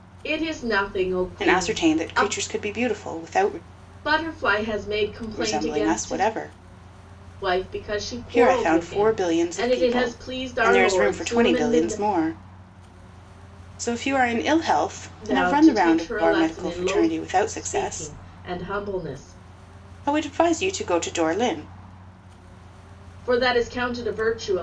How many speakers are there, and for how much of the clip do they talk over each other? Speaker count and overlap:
2, about 31%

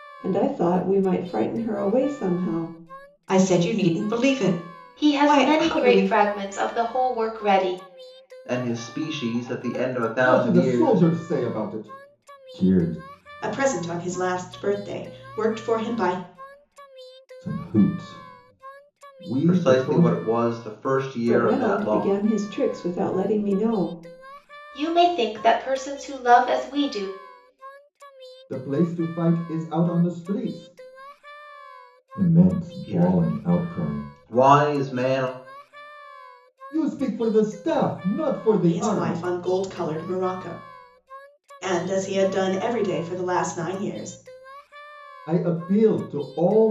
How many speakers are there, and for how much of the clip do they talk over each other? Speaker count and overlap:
6, about 12%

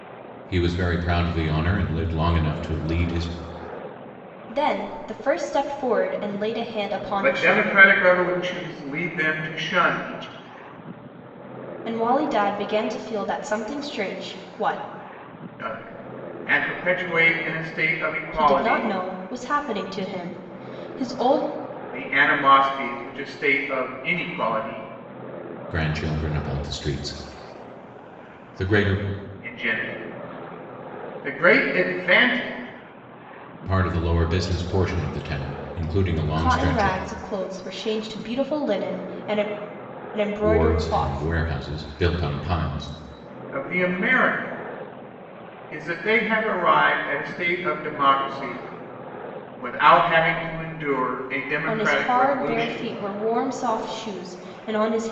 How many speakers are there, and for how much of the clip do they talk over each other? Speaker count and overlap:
3, about 8%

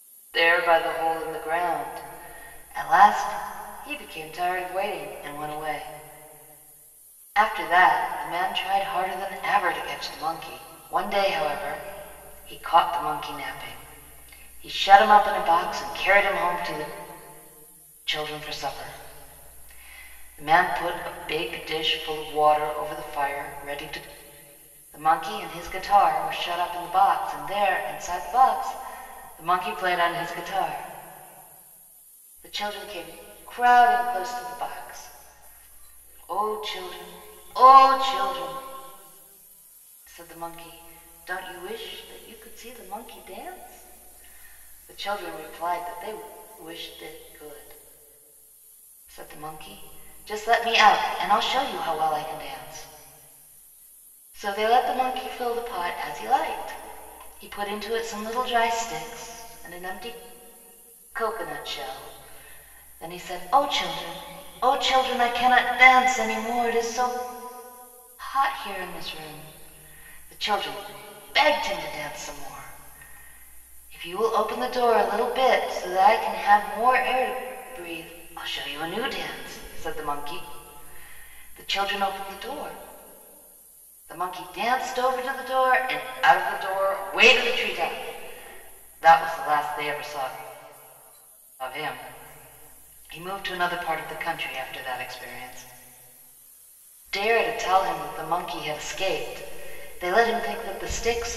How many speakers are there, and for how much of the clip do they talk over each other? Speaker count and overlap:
1, no overlap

